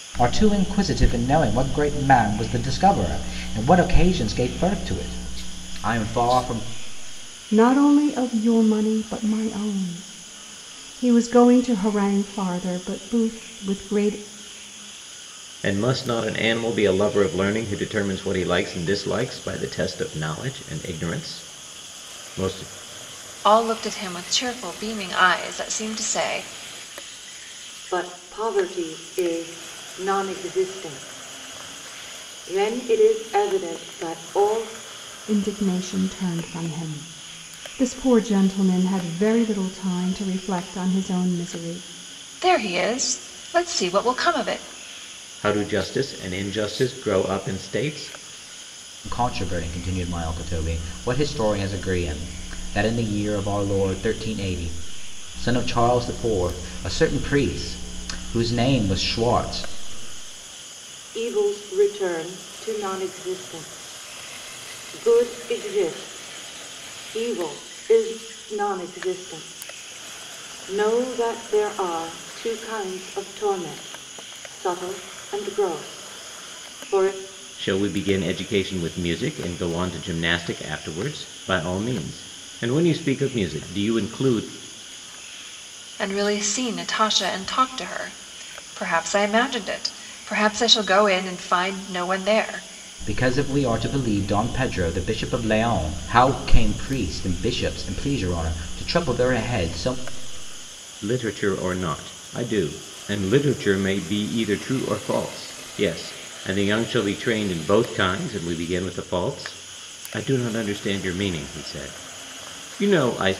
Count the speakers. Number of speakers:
5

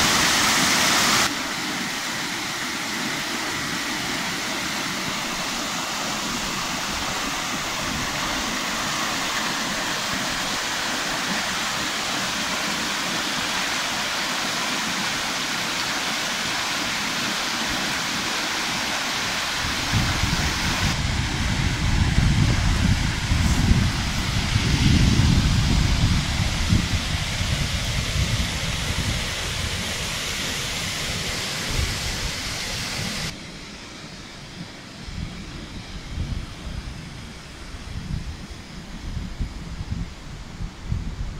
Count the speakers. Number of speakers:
0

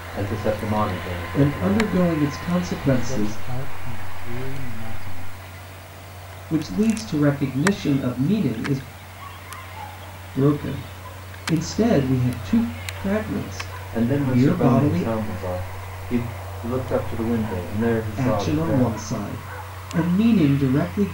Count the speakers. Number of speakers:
3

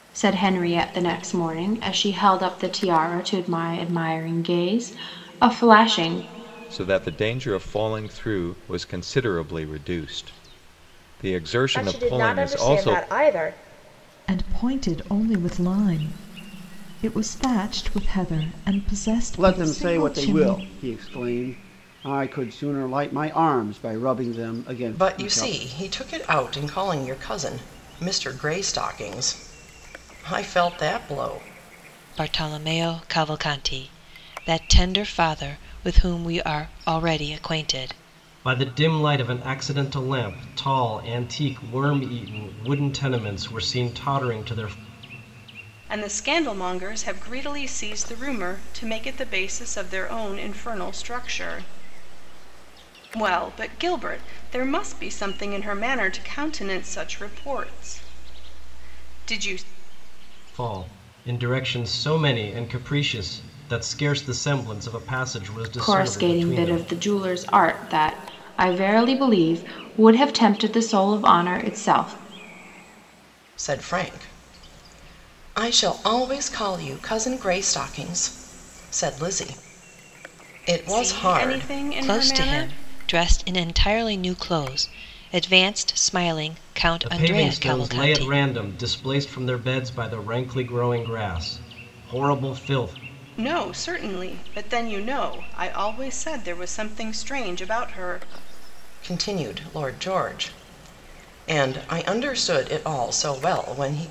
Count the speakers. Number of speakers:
9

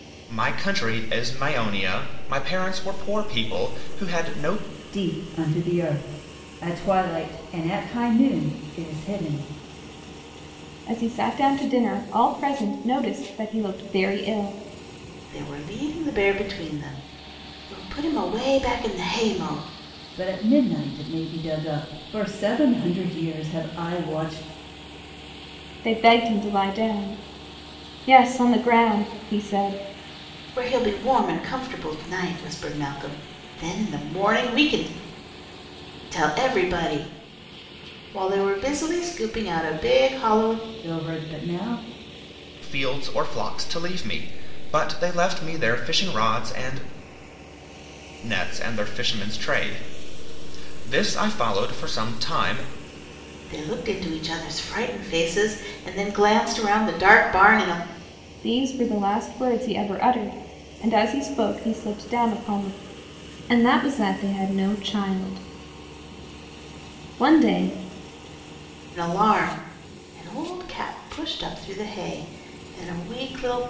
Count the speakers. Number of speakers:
4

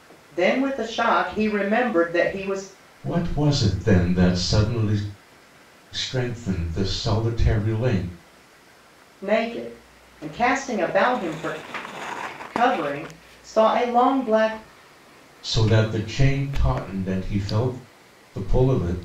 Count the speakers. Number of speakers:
2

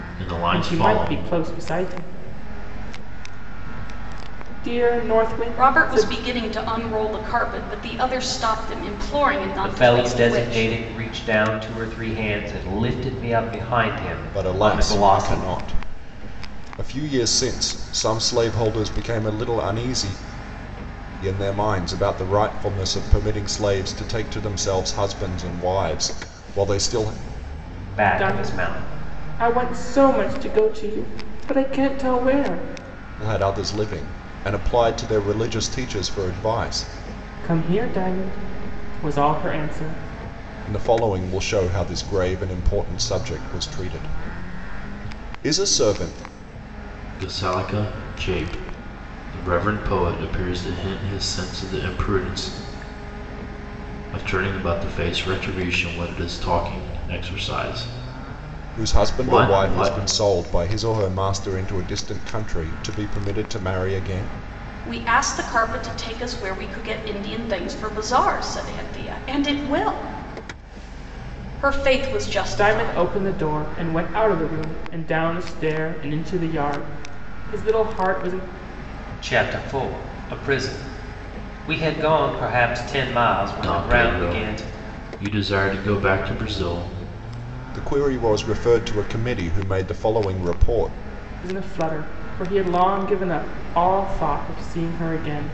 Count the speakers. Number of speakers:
5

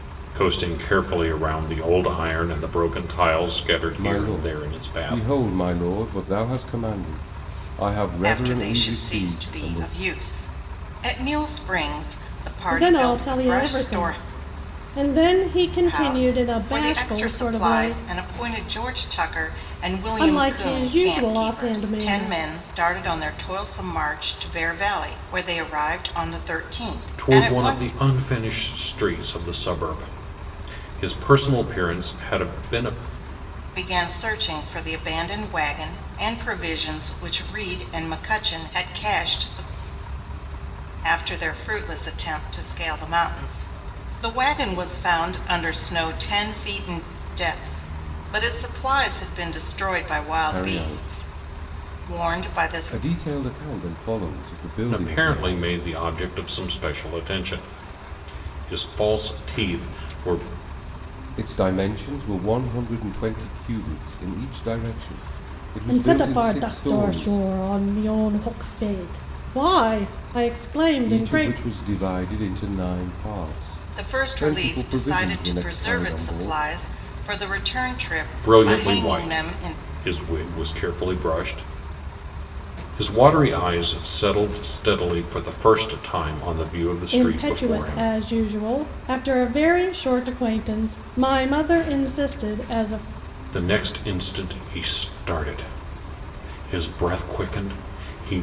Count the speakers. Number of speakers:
4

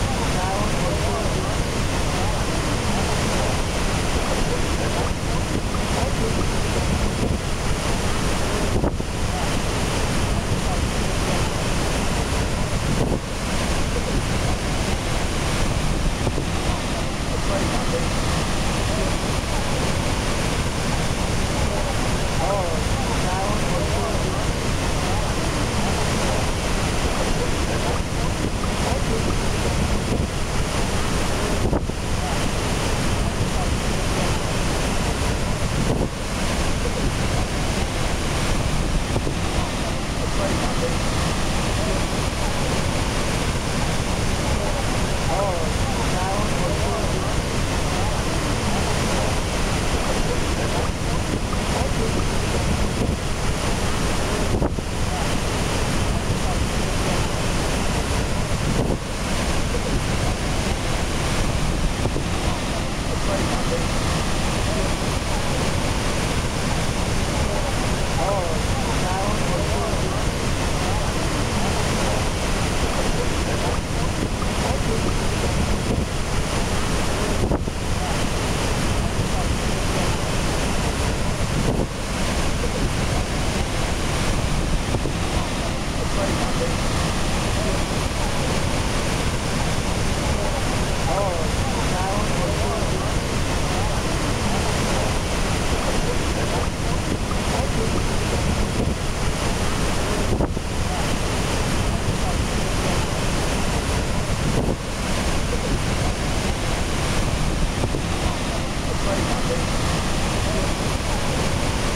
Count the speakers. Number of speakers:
0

